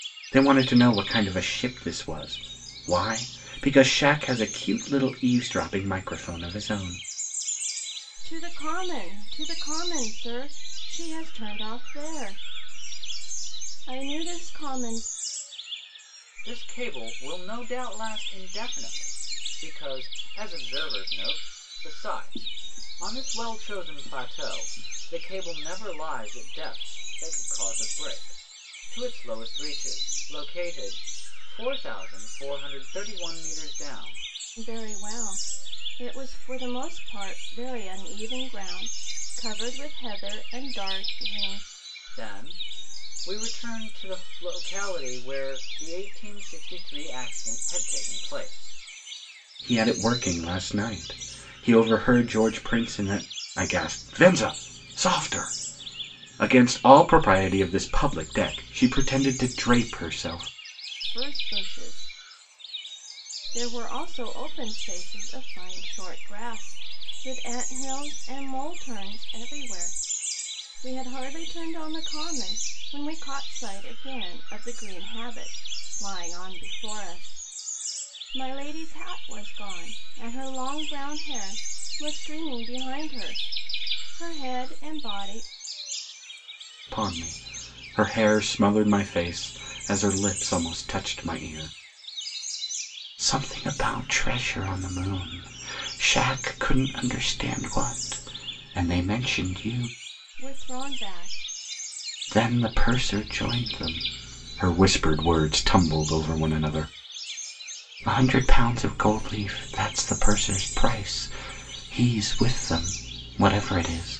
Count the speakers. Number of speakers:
three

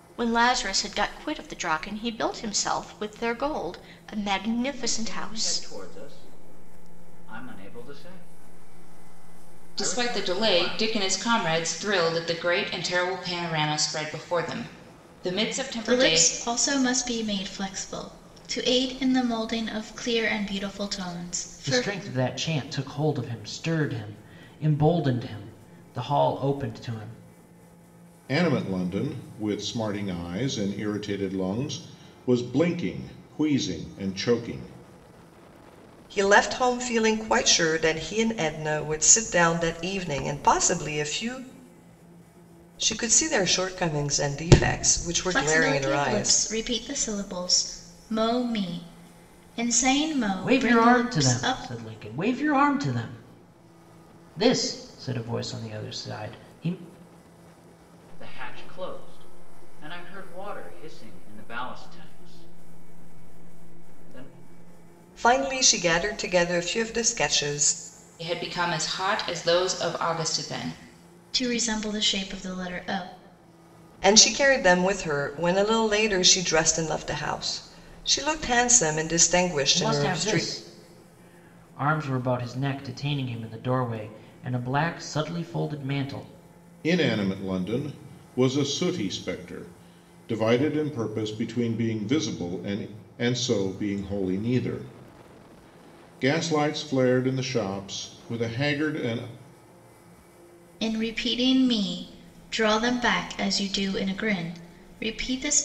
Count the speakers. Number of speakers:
seven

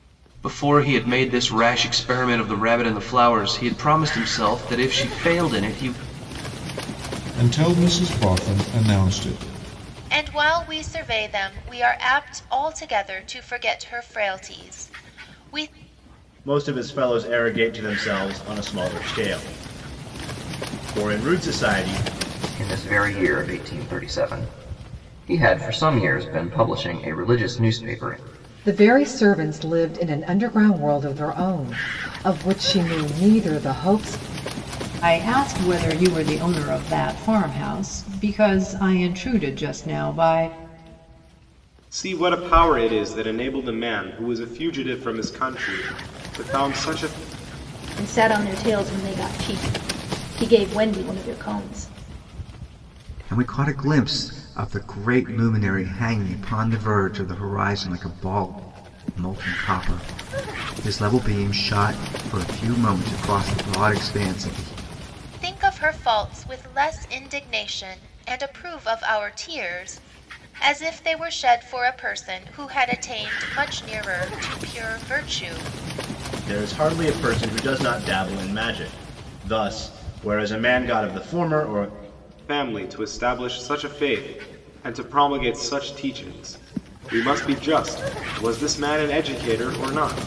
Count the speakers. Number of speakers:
ten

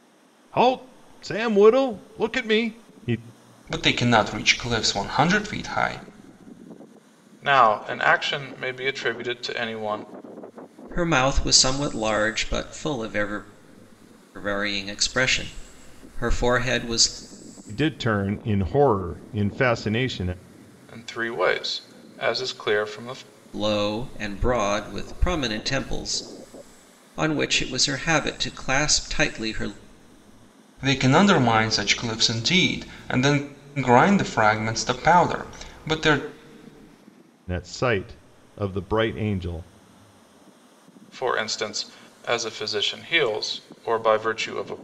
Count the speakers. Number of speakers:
four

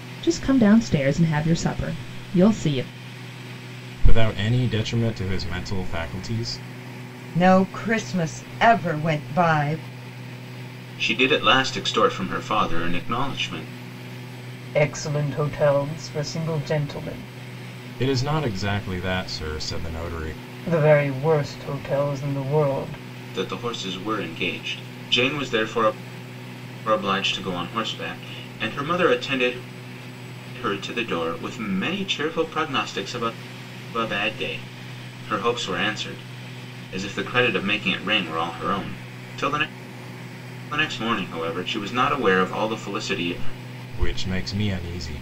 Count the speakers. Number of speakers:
five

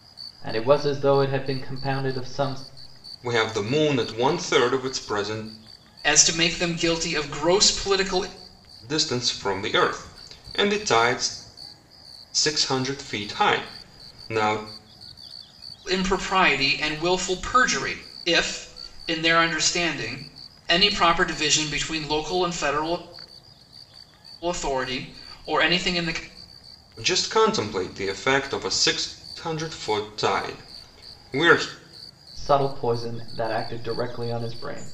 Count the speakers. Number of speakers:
three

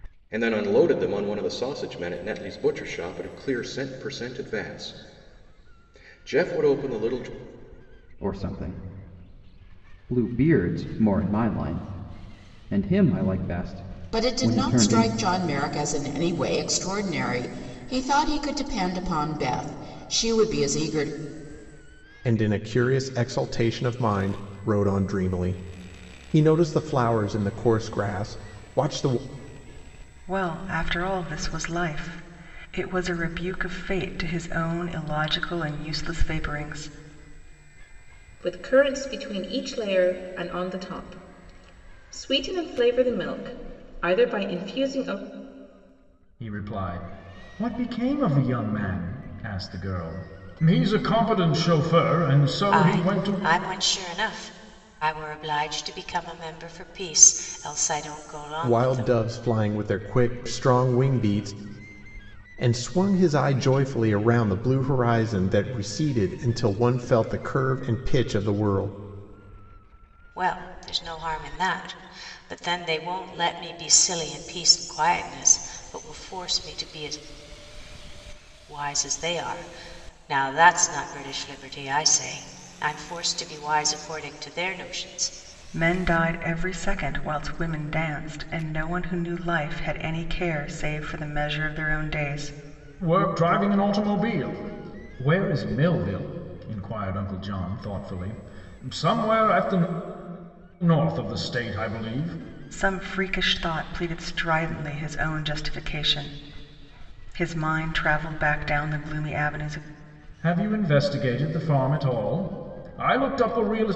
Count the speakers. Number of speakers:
eight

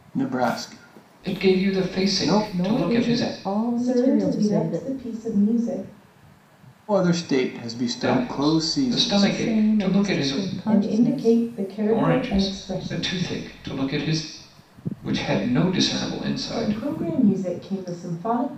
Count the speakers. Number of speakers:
four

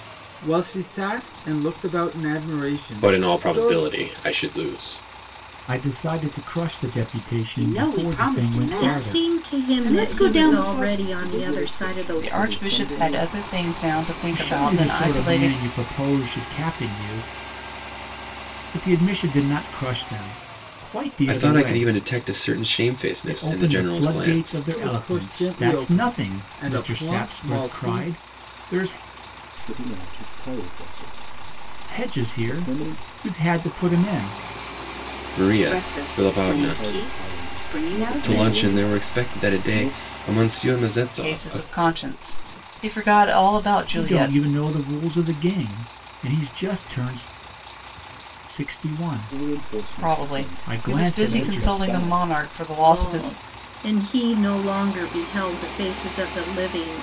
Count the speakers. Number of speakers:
seven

